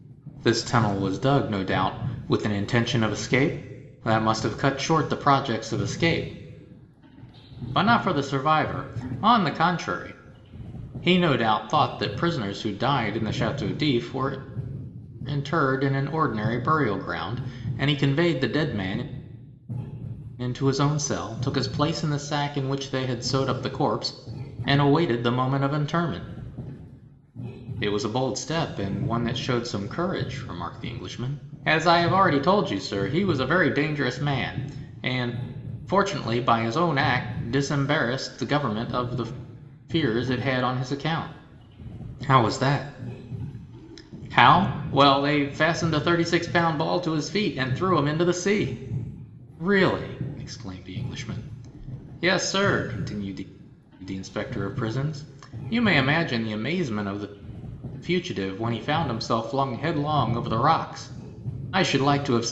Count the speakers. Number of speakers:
1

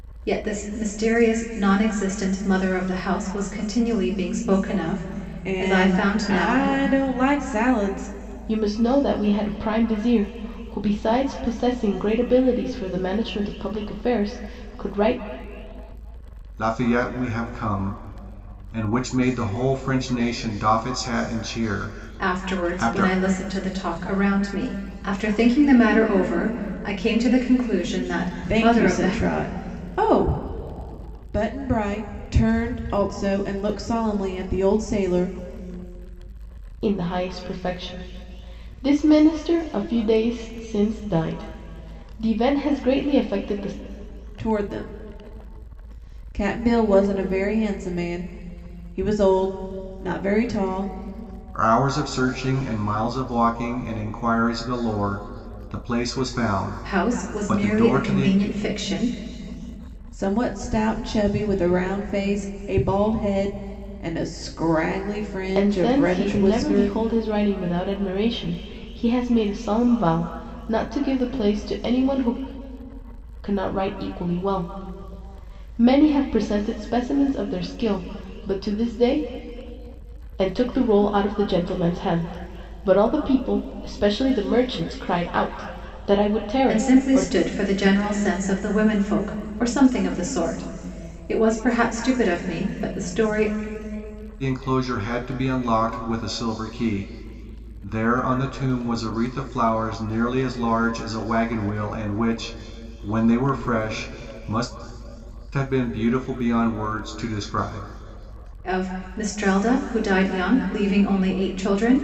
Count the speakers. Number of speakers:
4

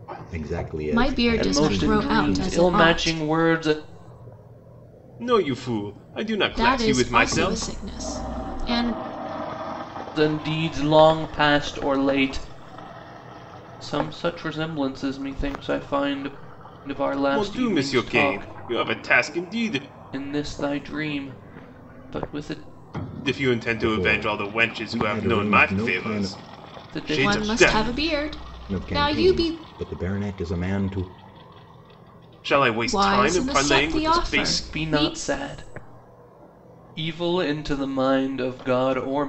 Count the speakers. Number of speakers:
4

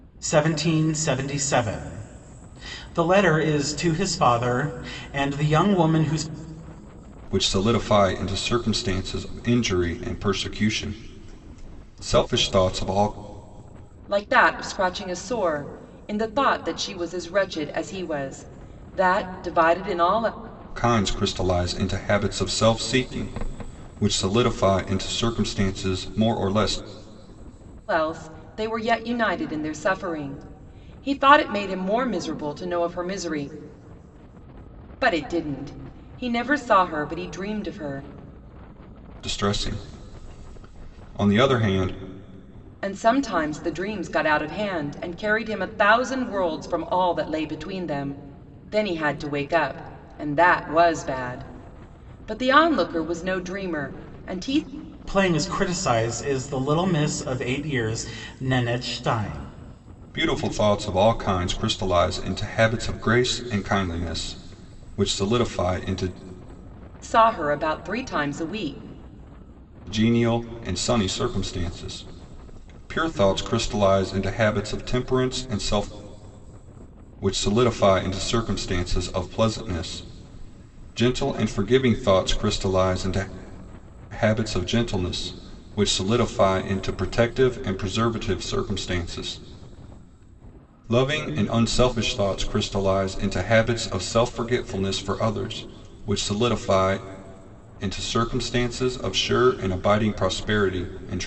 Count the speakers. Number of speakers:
3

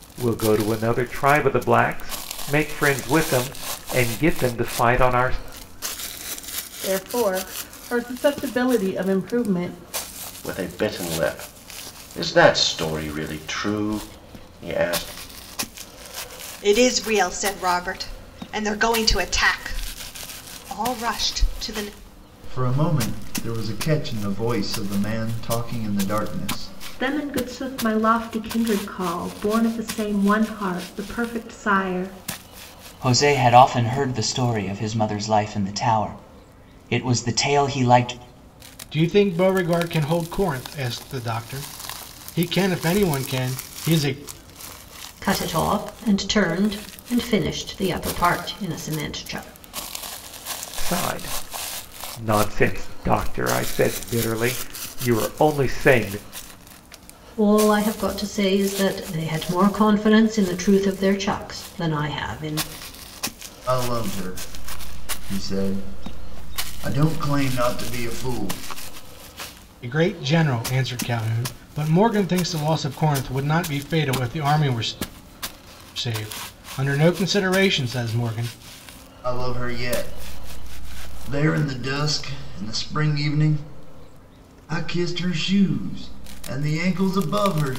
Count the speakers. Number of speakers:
9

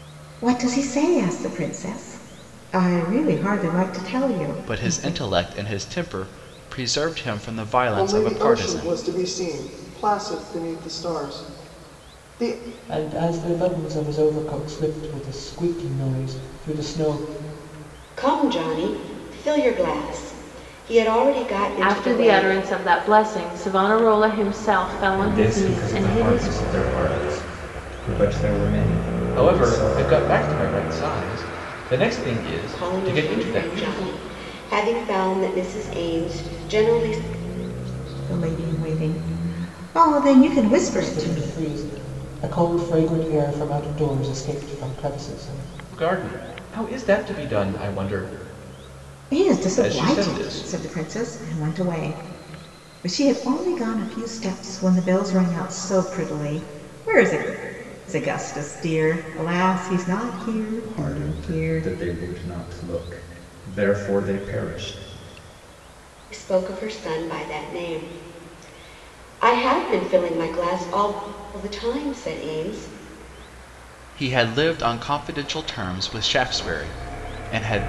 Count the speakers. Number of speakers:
8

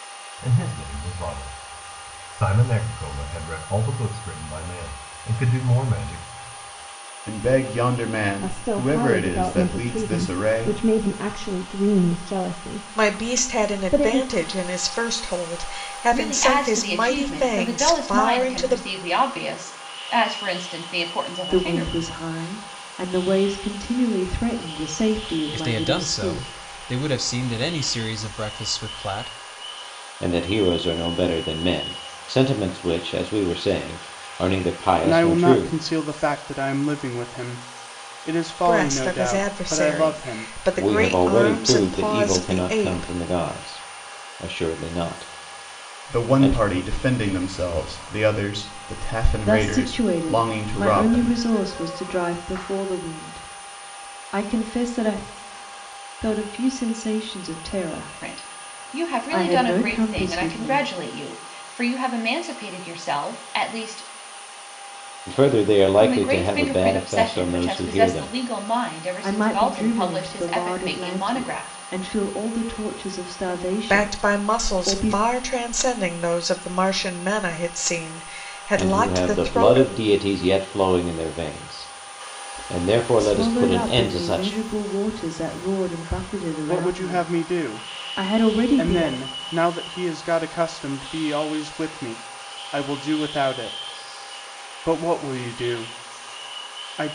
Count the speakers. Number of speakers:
9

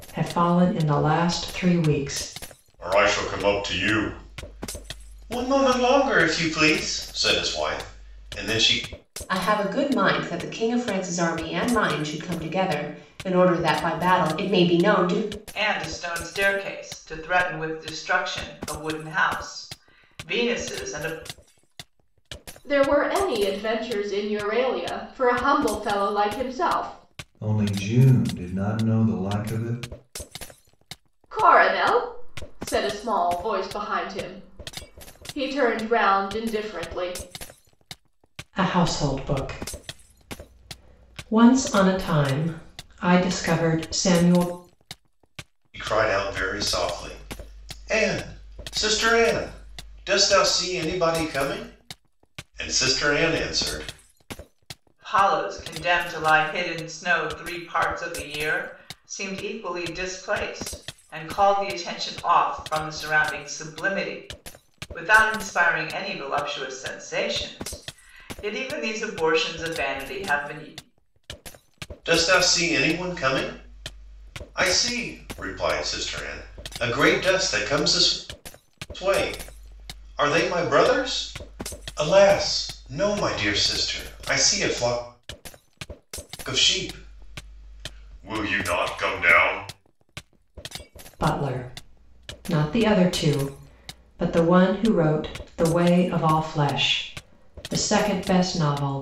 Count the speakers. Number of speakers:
6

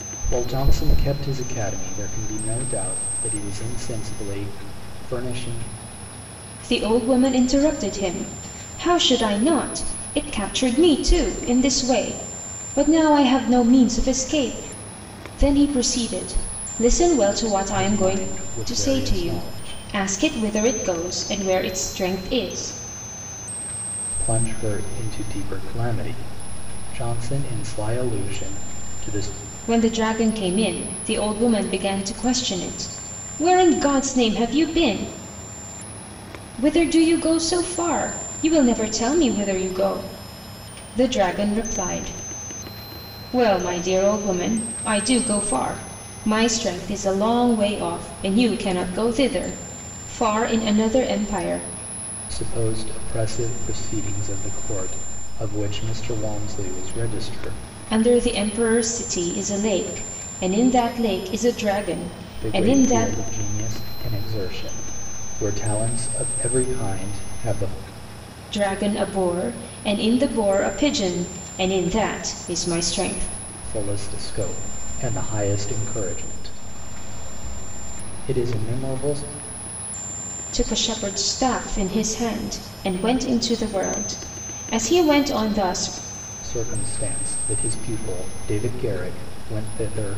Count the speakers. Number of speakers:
2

